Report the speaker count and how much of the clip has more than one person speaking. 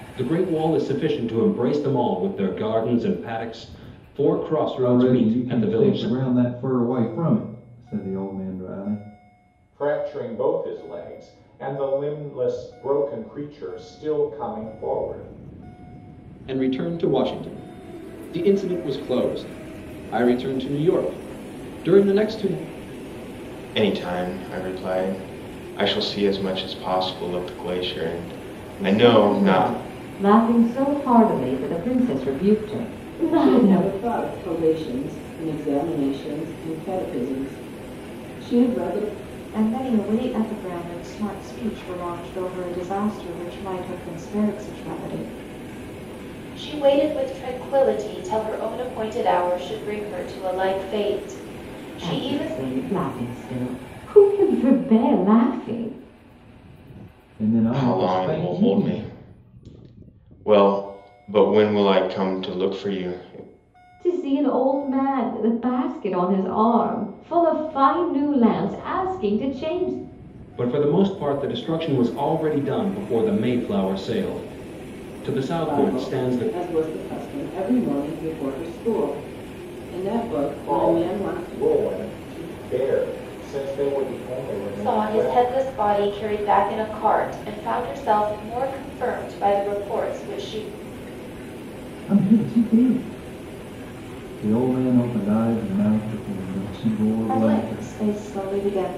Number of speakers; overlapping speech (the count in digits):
9, about 9%